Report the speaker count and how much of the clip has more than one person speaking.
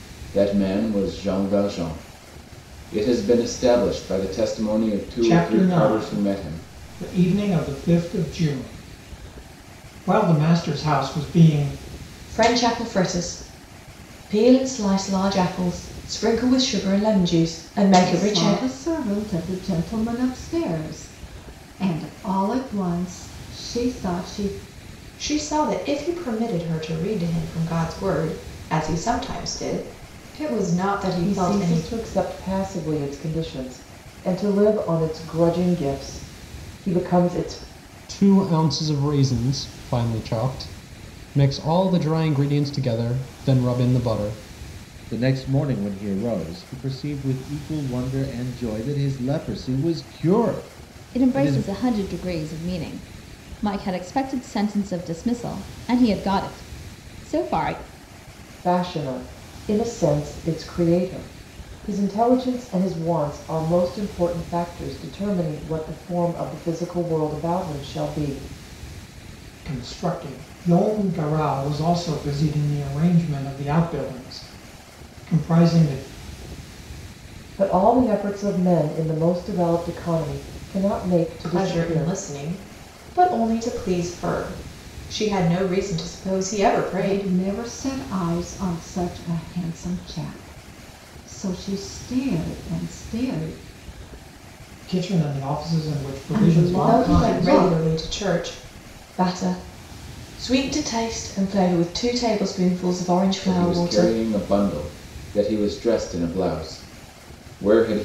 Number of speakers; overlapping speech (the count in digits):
9, about 6%